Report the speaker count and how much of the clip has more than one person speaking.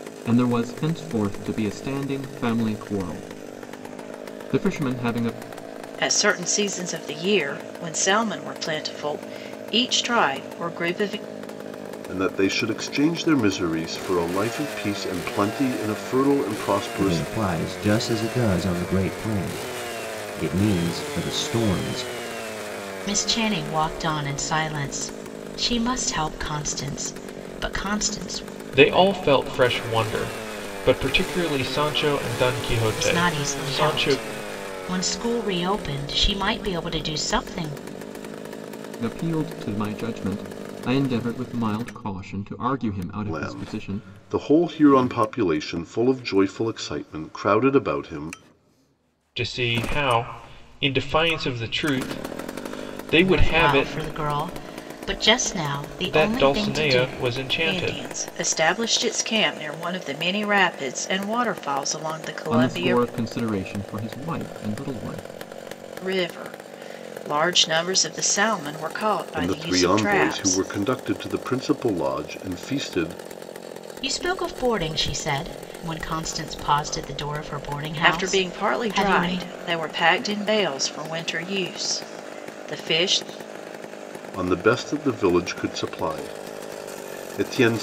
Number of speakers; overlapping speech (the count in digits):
6, about 9%